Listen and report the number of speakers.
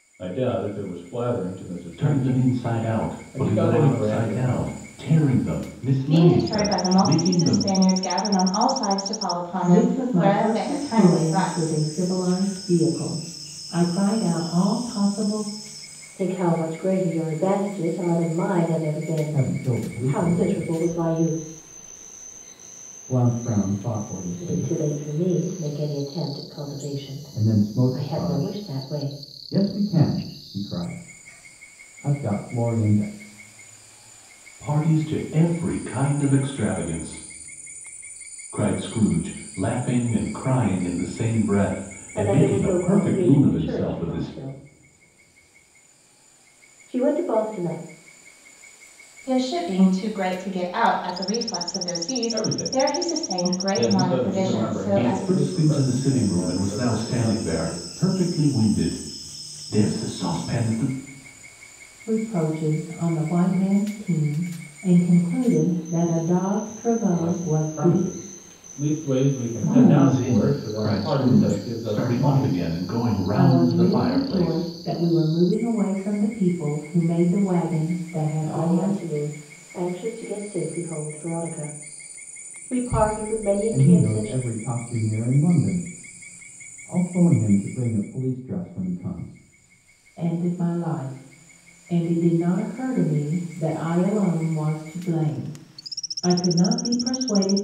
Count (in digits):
6